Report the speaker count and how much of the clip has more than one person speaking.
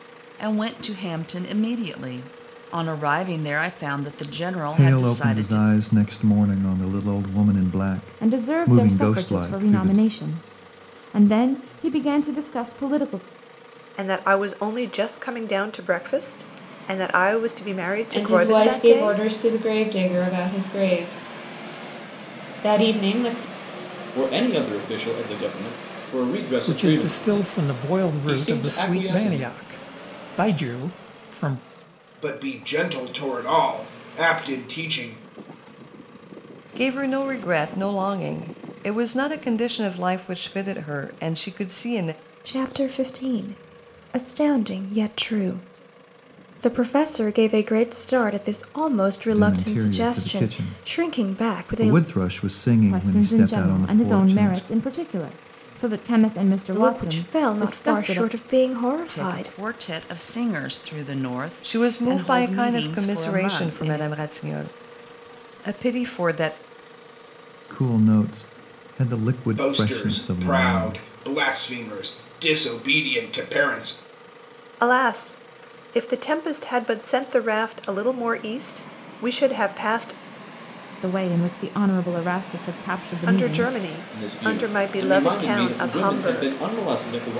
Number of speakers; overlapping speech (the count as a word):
ten, about 23%